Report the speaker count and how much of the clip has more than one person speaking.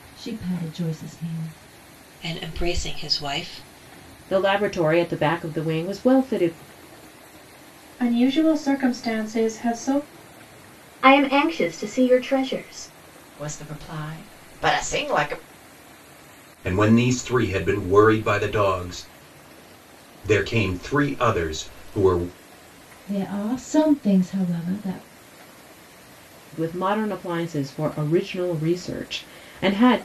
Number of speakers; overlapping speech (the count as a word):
seven, no overlap